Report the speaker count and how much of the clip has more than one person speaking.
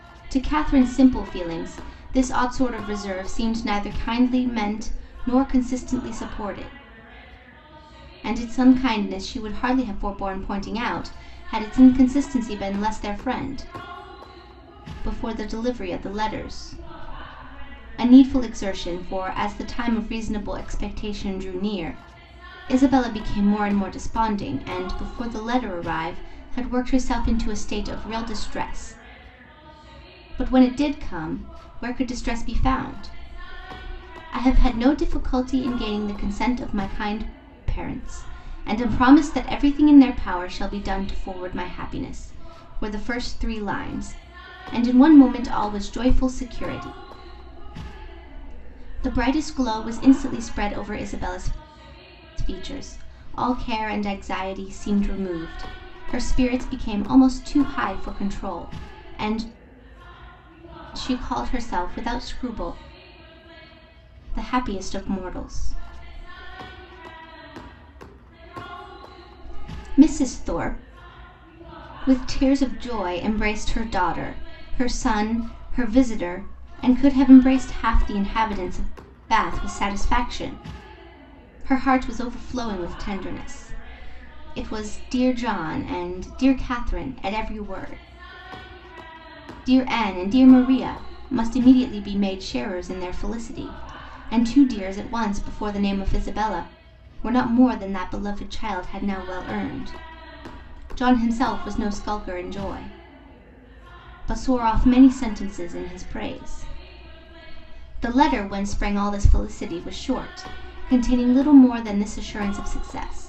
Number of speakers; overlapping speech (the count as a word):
one, no overlap